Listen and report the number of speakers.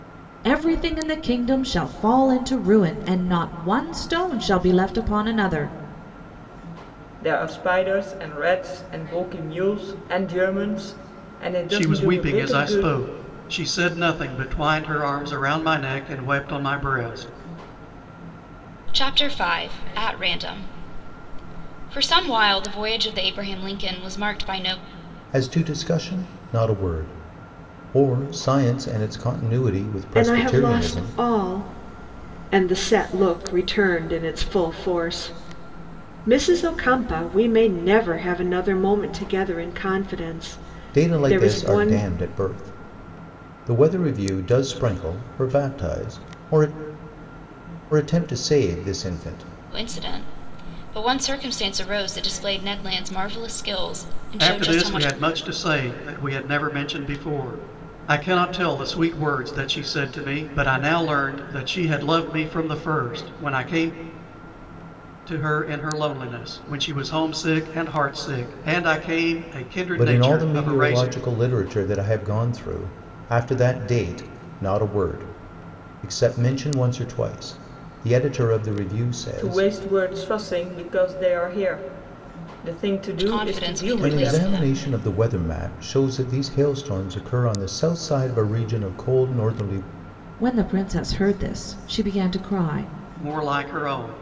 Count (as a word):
six